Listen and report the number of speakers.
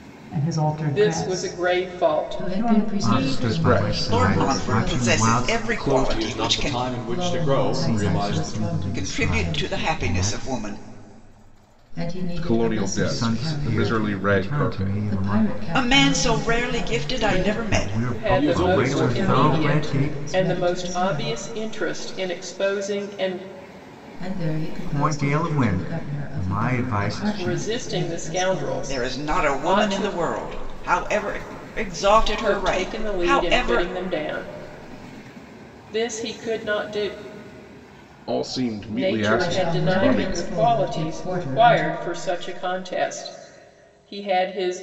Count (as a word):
seven